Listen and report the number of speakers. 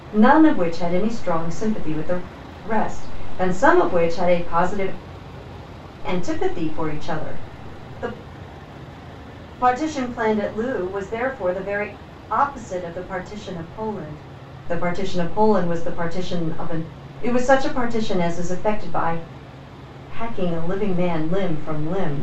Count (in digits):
1